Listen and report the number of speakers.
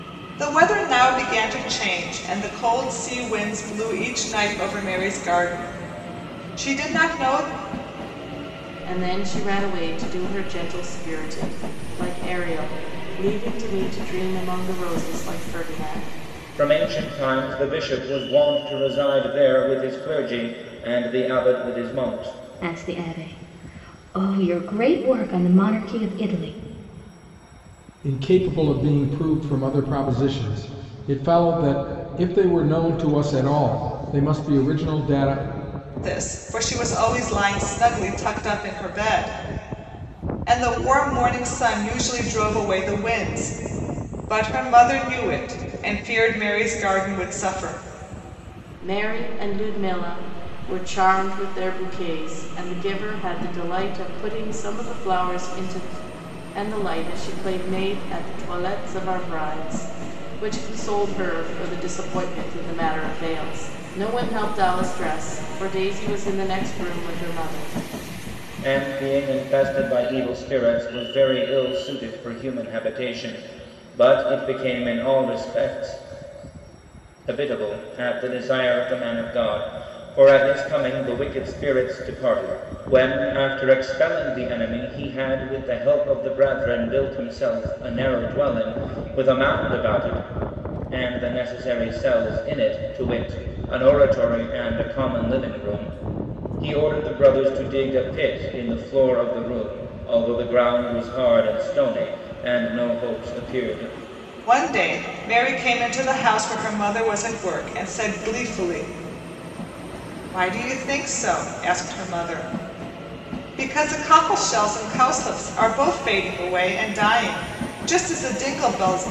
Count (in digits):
5